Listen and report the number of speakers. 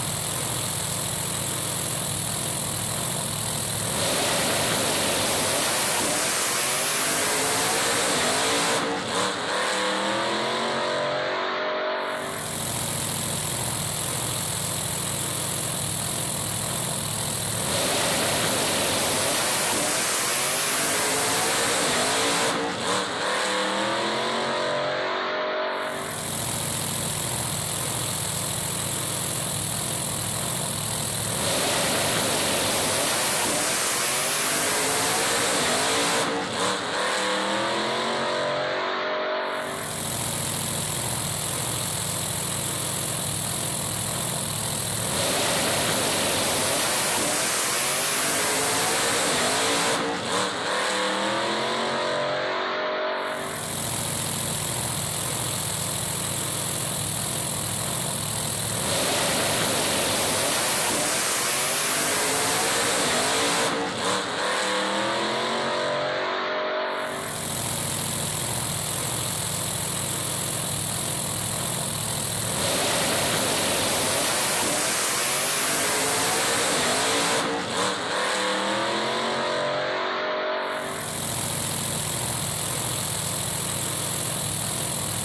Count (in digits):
0